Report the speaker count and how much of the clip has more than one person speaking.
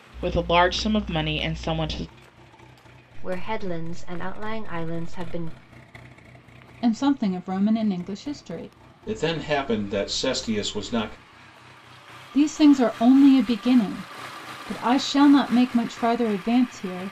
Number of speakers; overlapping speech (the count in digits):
4, no overlap